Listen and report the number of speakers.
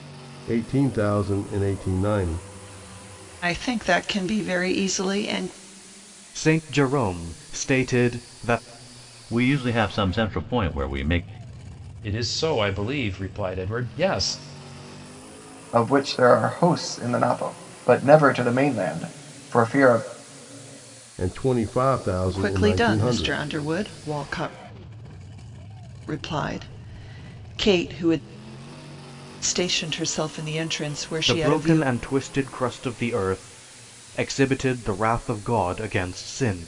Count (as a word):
six